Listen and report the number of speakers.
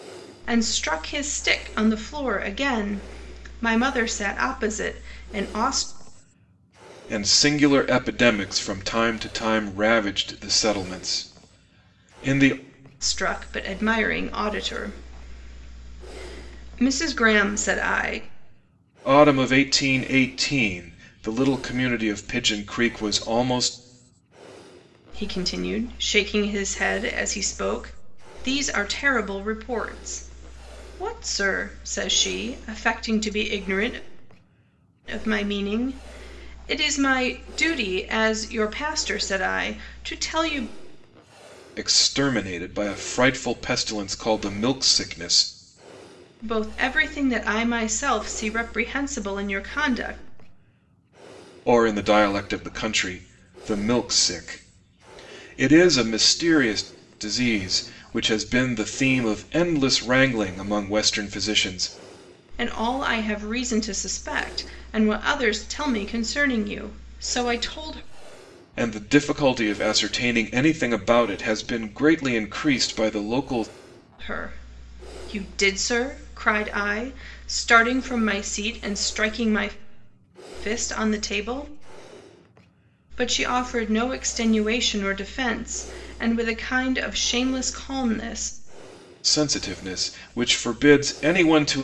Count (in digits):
2